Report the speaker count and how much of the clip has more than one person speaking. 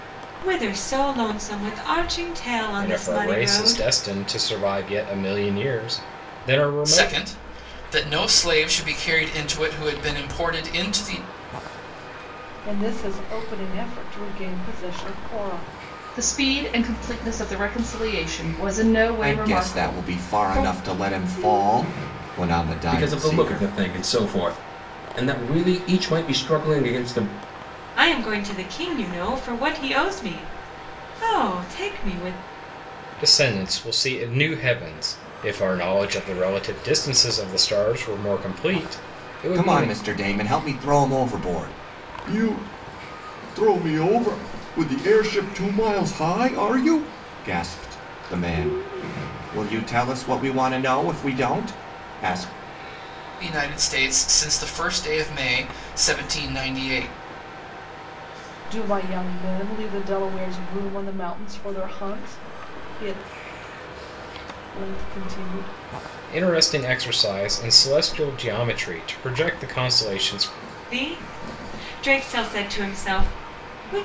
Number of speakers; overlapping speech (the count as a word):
seven, about 6%